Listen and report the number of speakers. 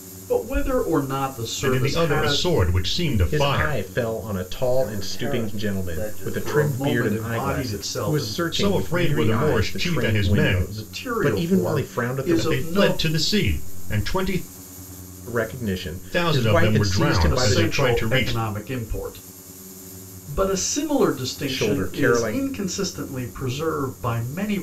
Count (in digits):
4